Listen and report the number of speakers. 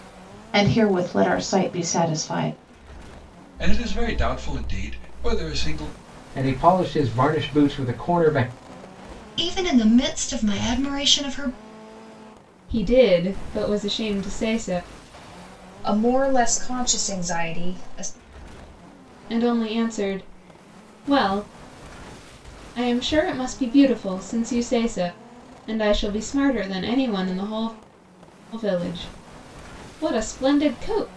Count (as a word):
six